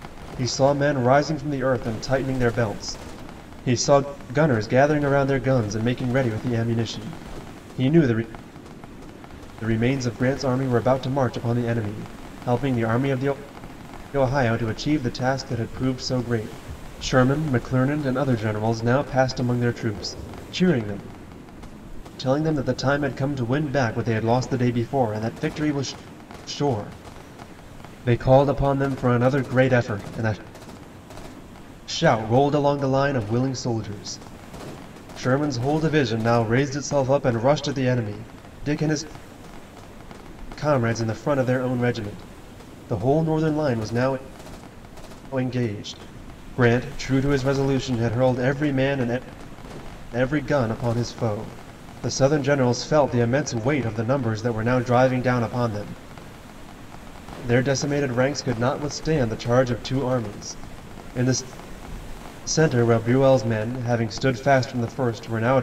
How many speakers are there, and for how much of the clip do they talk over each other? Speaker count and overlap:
1, no overlap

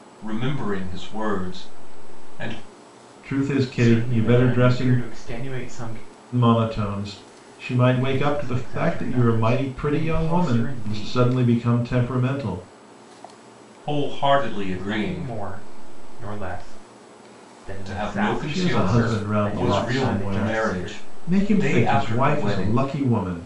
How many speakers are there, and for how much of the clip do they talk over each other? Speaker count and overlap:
3, about 42%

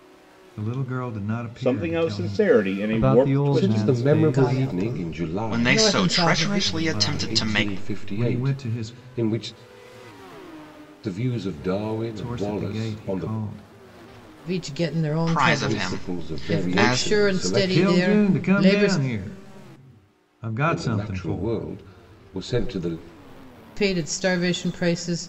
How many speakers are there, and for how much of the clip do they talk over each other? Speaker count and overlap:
6, about 52%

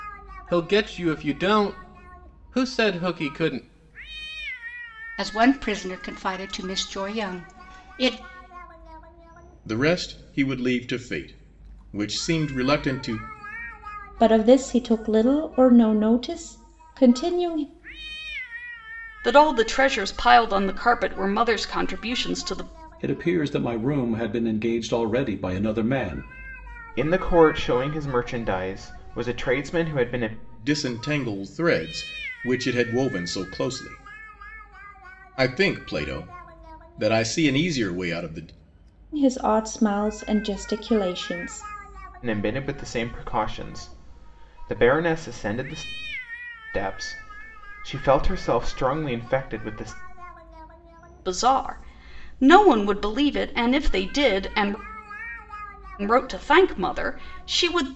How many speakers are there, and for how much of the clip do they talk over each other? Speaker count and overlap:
7, no overlap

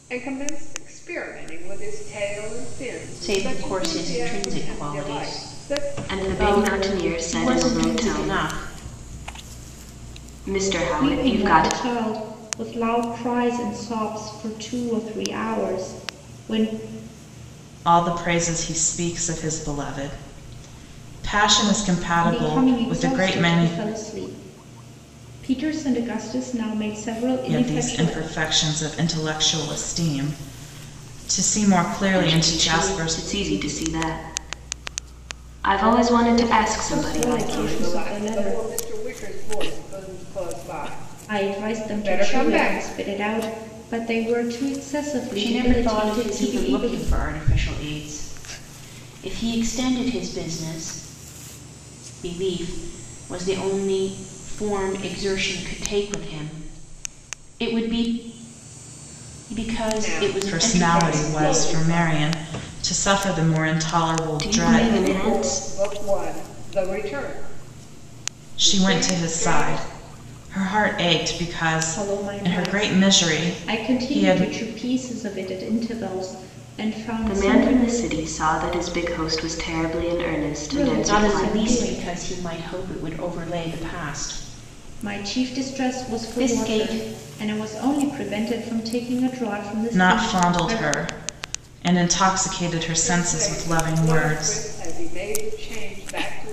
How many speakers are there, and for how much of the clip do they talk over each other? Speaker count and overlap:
5, about 30%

